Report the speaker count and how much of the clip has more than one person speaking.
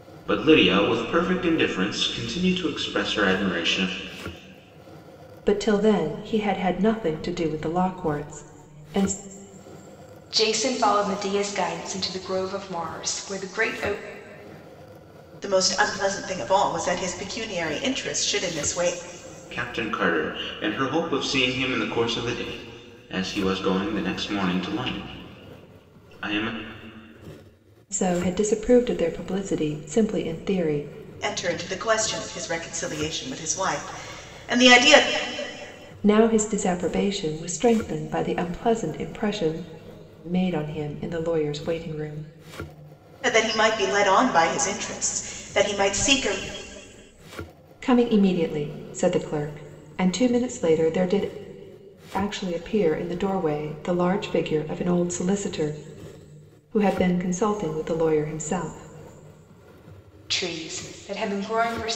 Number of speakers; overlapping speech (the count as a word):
four, no overlap